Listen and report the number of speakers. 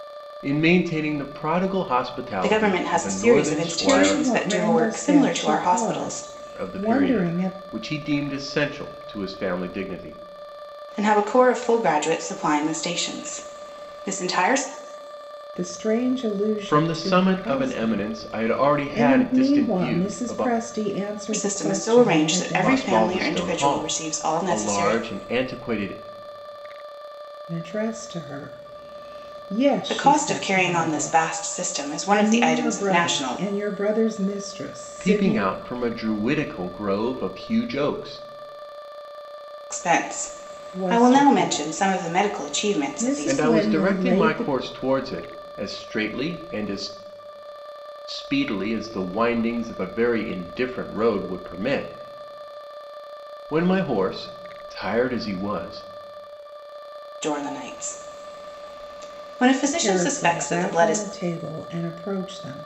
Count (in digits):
3